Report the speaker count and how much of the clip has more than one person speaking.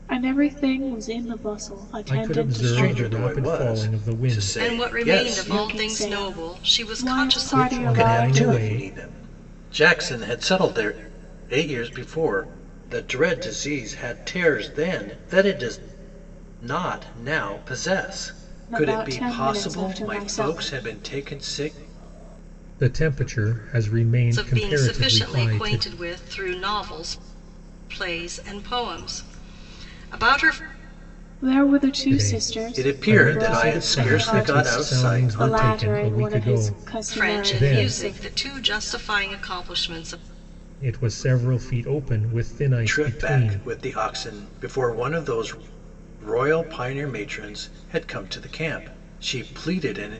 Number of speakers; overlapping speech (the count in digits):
4, about 34%